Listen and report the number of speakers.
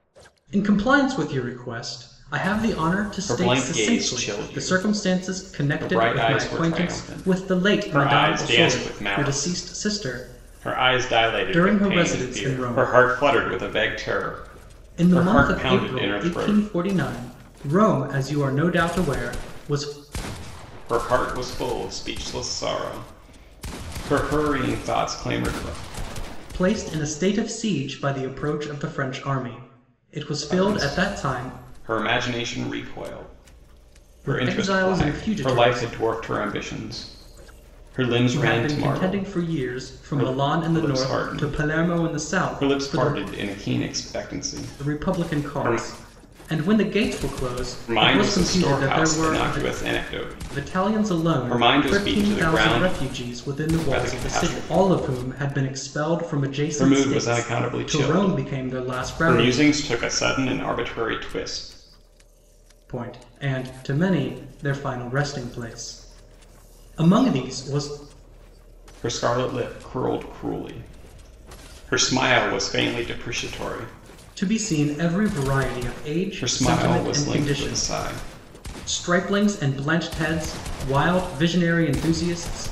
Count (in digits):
2